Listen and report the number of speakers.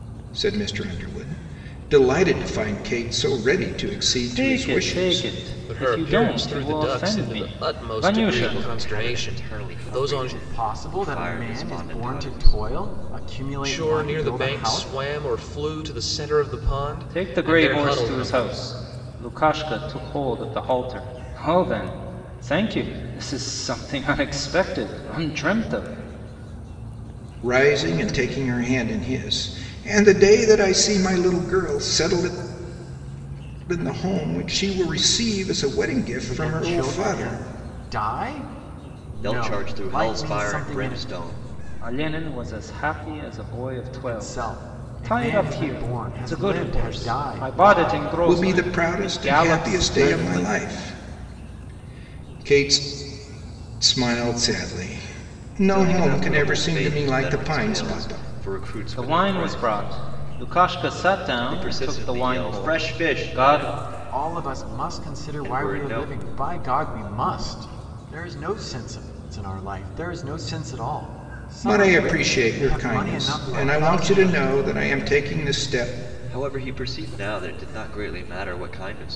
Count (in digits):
5